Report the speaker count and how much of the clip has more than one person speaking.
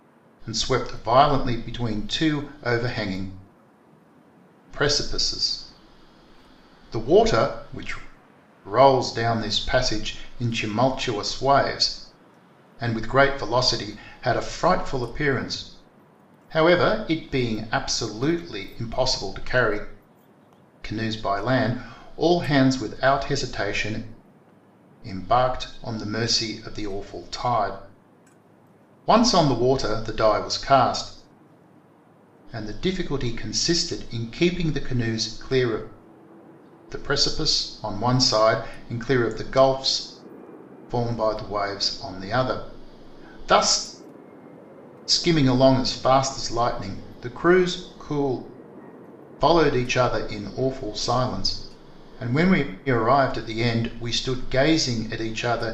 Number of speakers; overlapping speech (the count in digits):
1, no overlap